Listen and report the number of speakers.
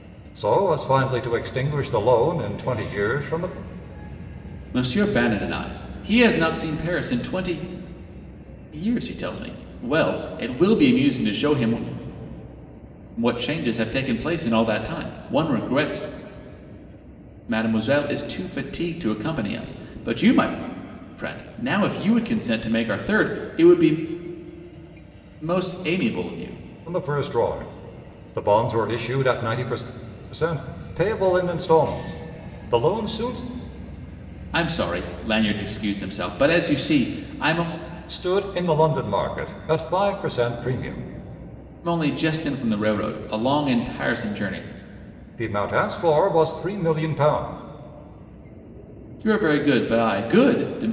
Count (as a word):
two